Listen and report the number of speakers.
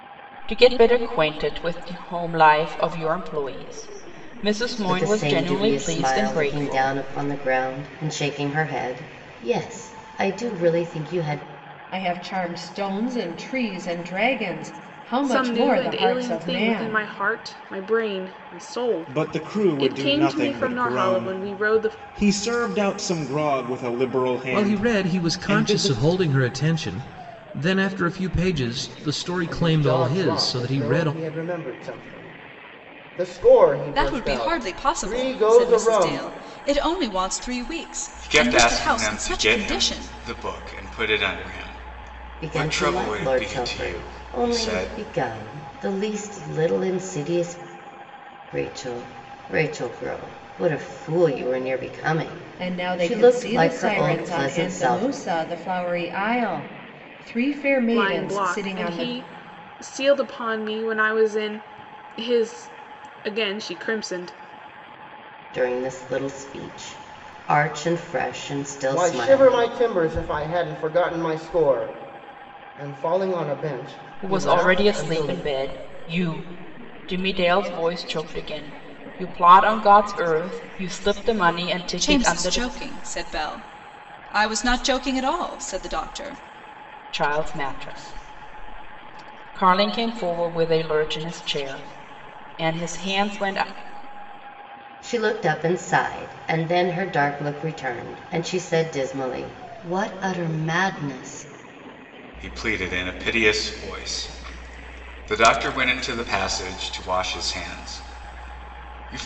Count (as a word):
nine